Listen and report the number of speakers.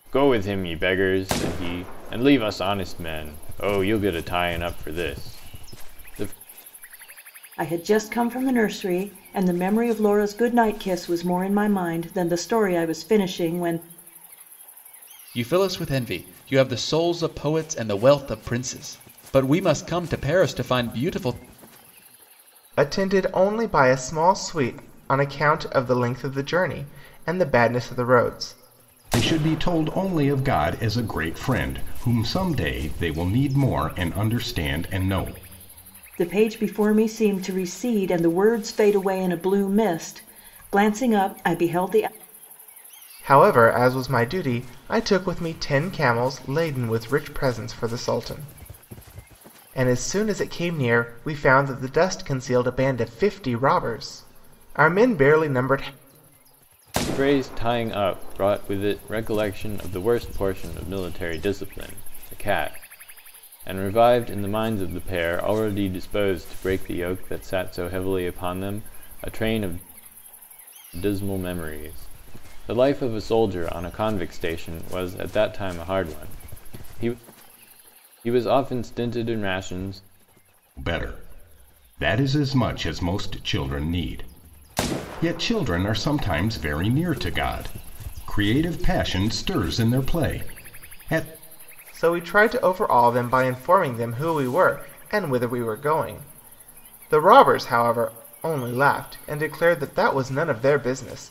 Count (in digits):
5